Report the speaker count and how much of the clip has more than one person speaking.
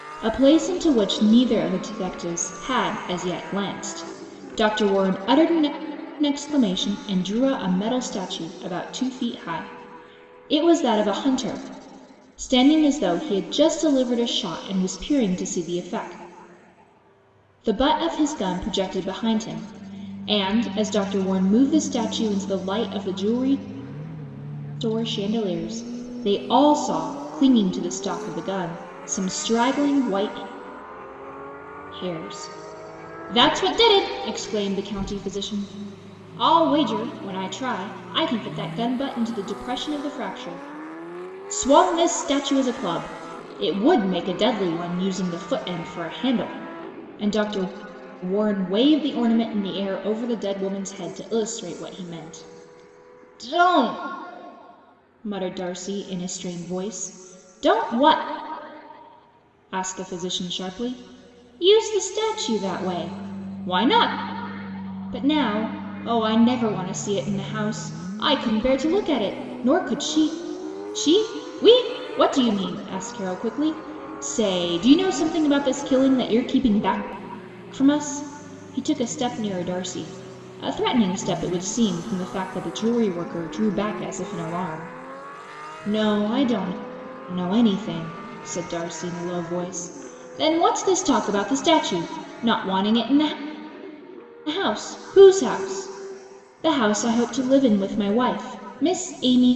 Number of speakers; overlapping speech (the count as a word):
one, no overlap